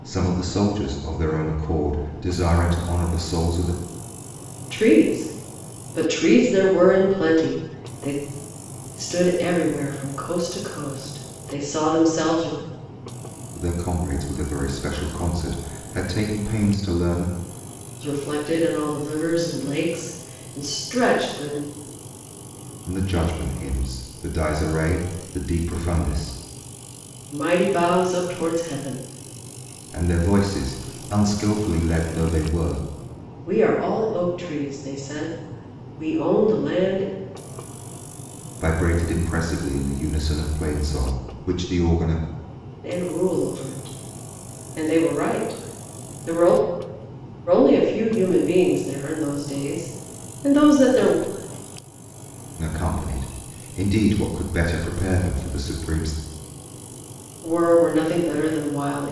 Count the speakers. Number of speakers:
2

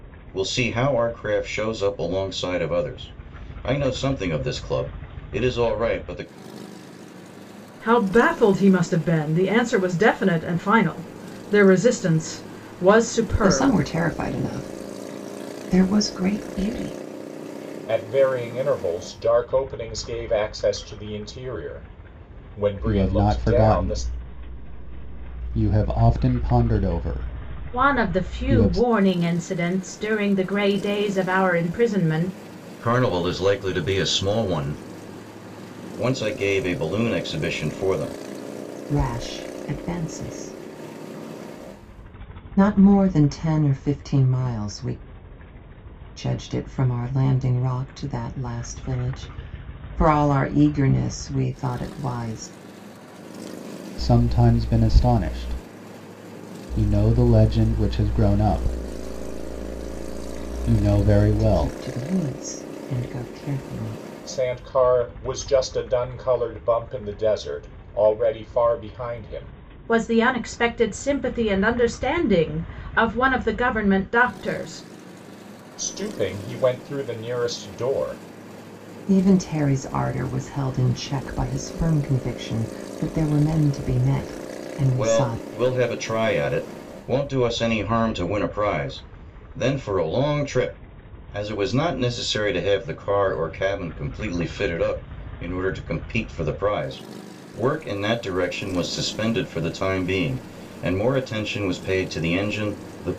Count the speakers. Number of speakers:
5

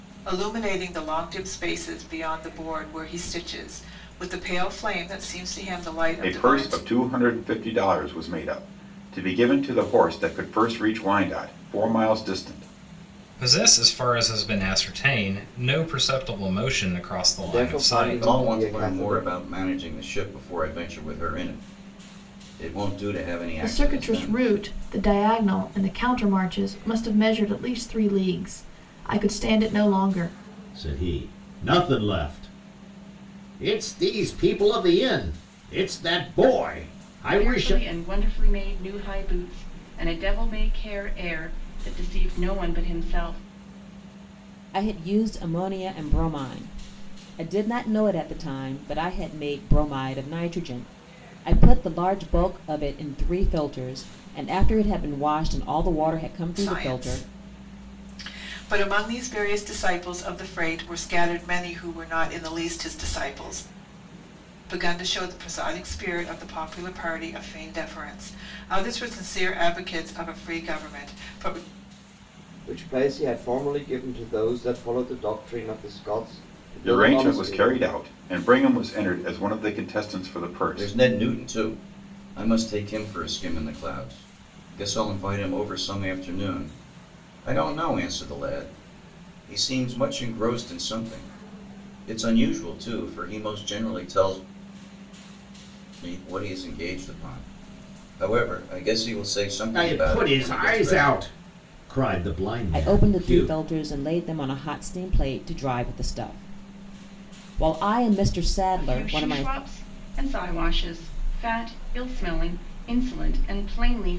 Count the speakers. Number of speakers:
9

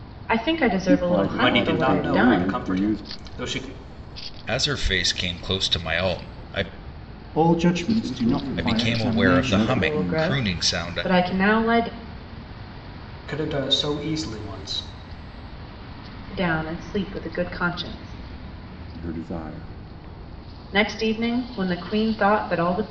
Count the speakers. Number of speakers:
5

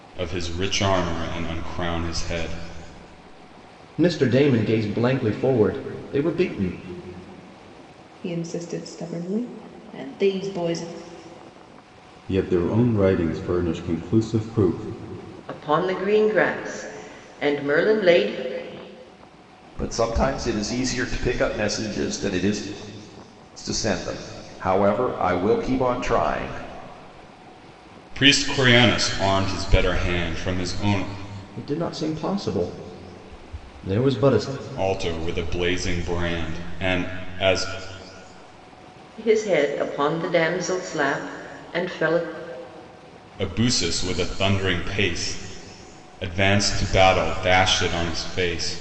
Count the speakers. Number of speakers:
6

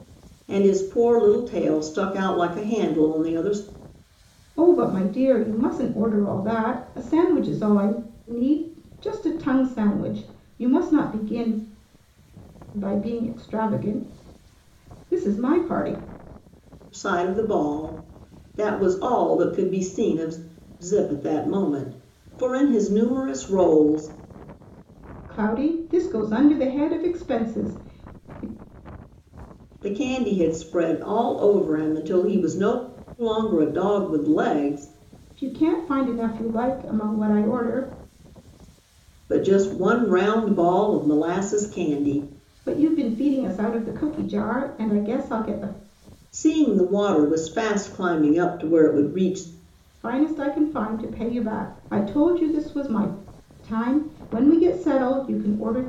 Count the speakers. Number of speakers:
2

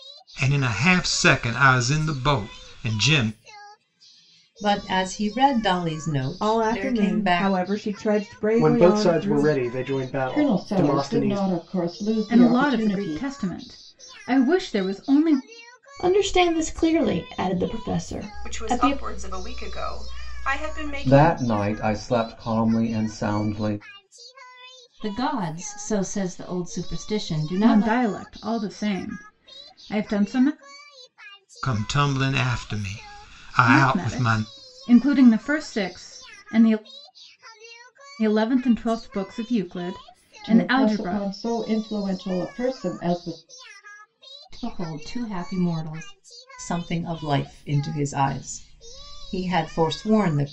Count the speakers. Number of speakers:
10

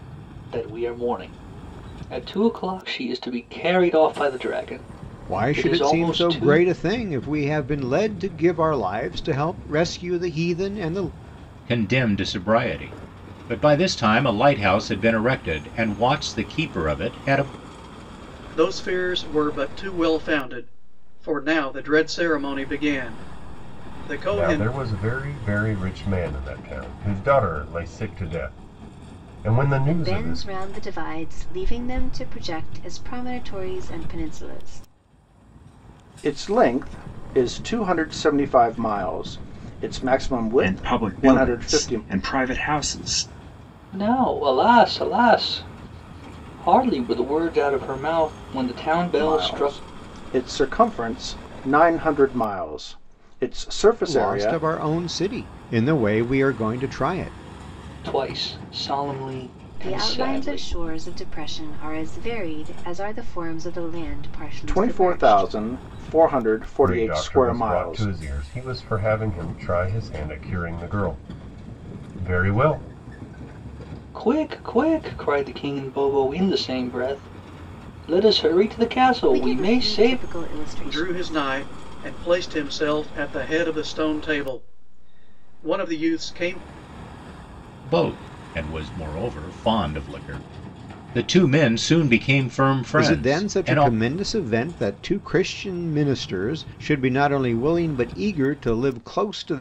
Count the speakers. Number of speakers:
8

